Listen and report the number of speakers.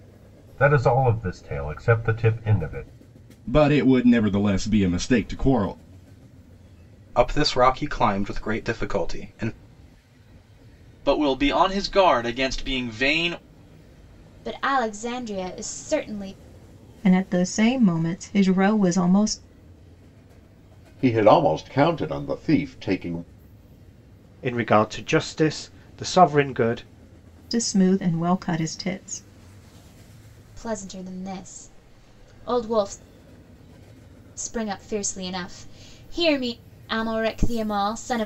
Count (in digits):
8